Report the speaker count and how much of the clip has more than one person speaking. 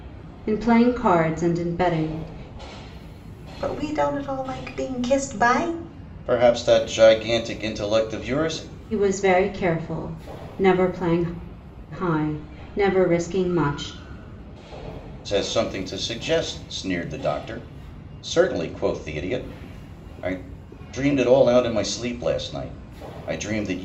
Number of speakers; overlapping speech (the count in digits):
3, no overlap